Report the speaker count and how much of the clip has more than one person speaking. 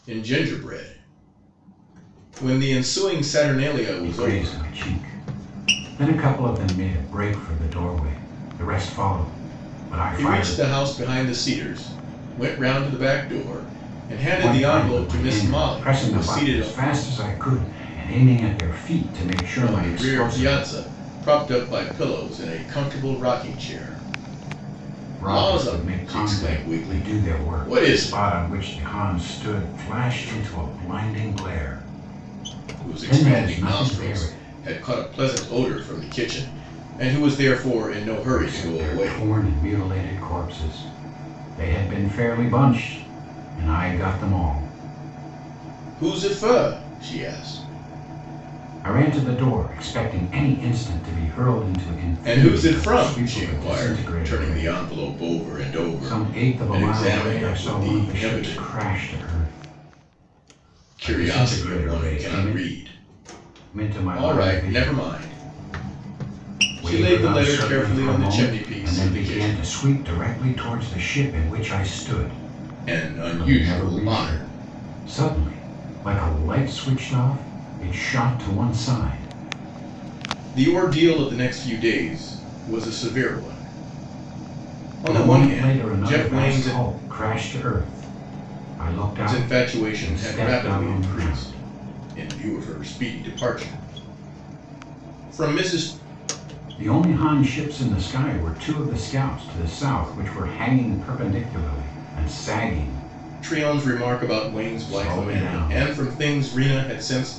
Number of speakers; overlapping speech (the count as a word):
two, about 25%